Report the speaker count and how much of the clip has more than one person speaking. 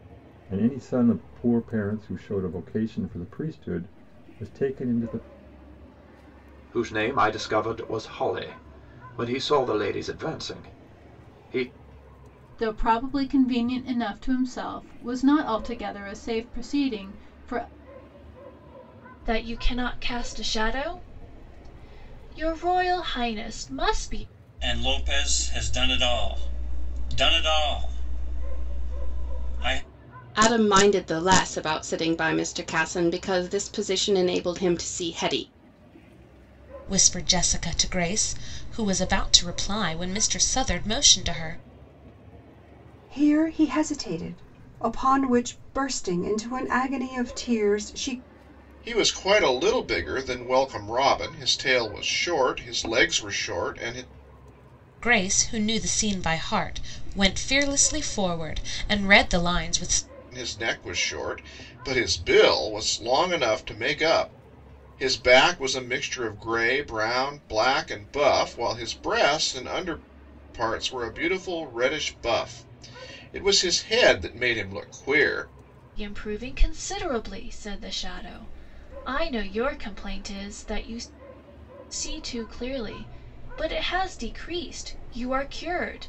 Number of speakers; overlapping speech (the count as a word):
nine, no overlap